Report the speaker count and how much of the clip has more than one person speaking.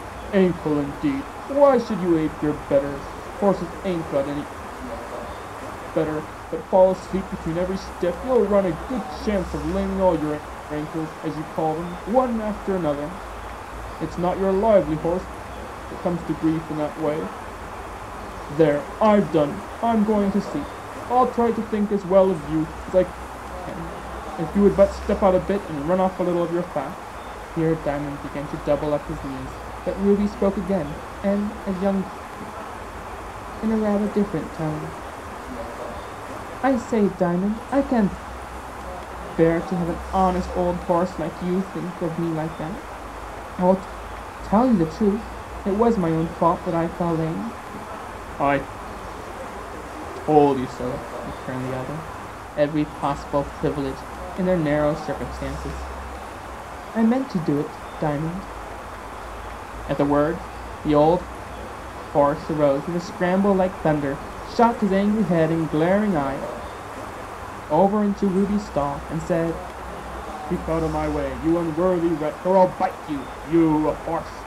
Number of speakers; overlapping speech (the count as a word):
one, no overlap